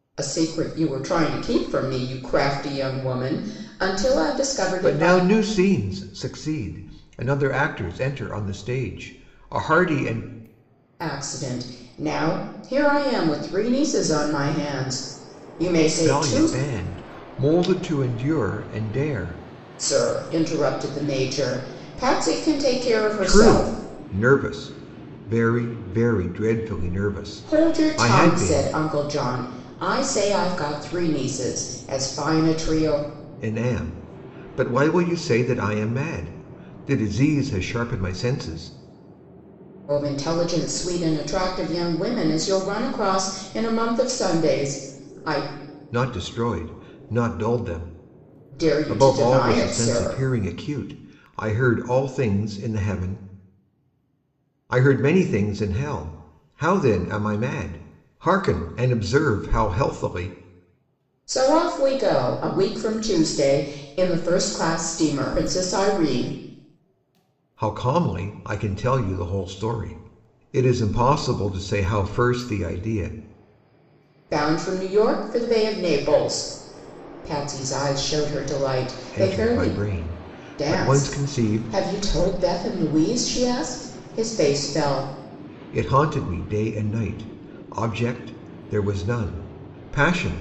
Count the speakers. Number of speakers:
two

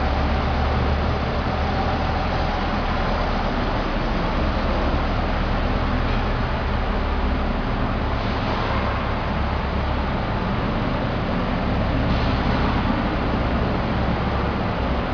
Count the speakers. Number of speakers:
zero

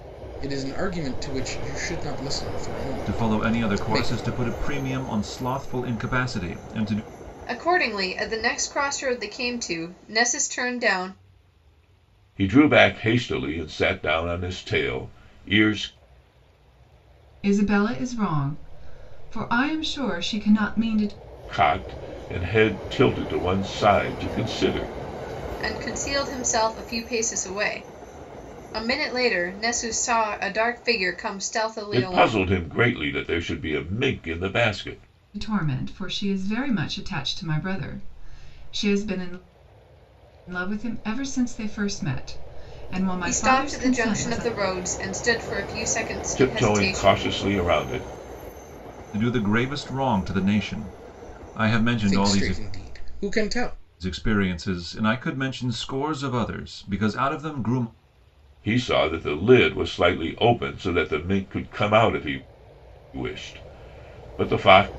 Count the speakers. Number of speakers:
five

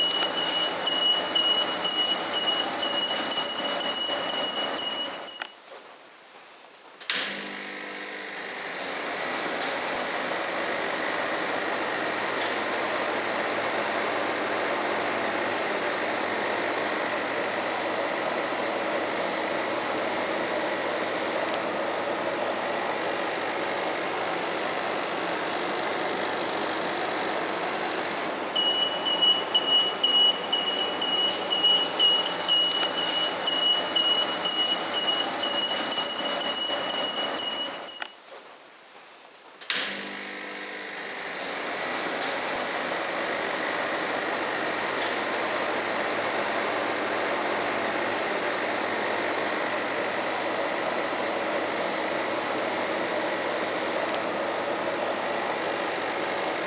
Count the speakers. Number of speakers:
zero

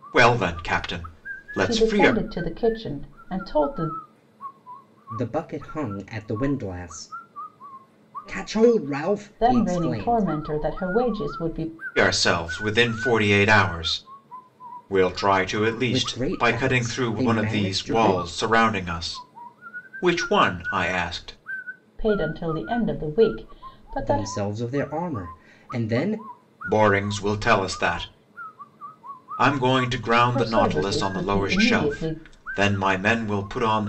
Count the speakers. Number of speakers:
three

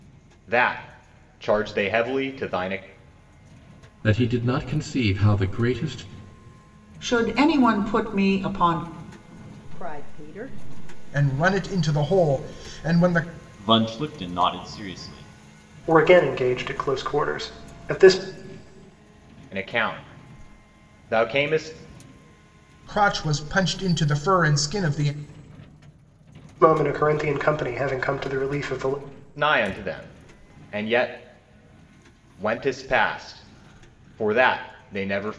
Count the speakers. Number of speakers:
seven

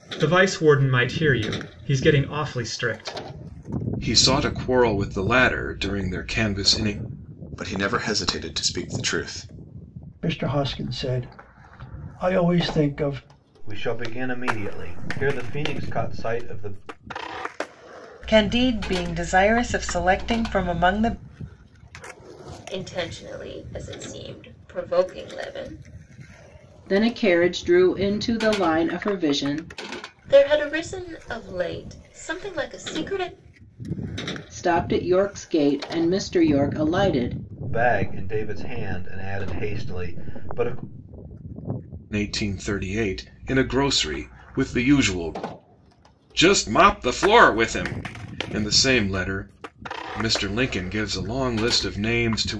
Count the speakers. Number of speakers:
eight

